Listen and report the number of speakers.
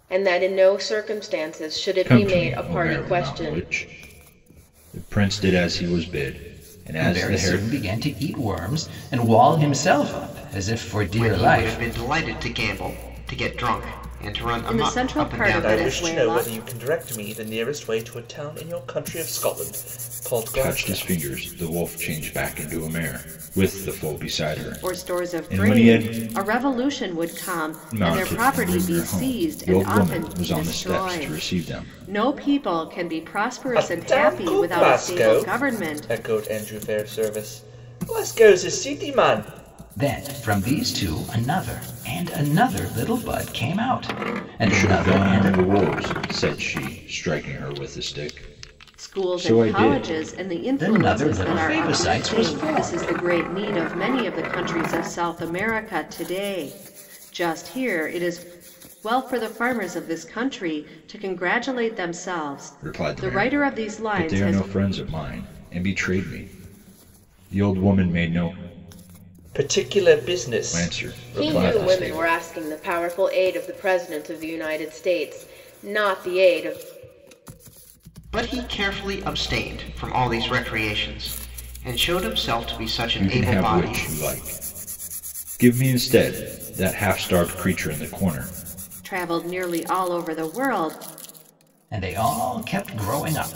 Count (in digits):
6